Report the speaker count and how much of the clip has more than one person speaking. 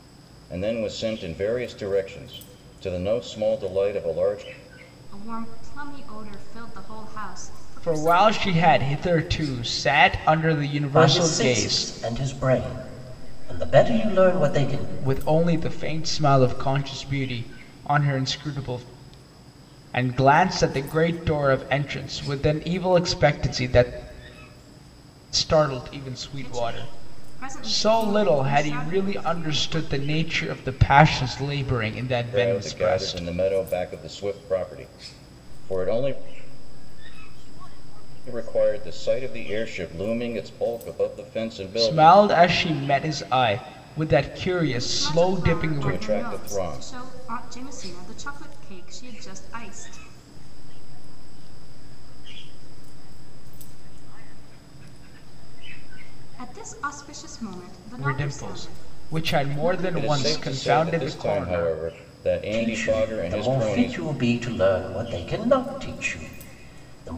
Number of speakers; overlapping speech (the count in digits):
5, about 34%